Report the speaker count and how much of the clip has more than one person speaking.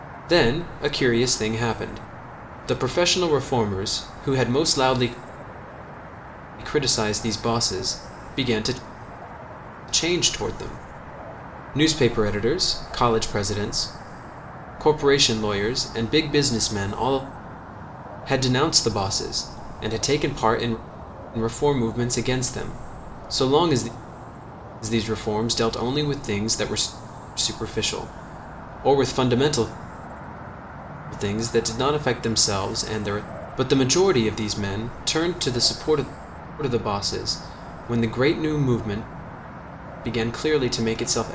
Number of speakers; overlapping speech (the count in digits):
1, no overlap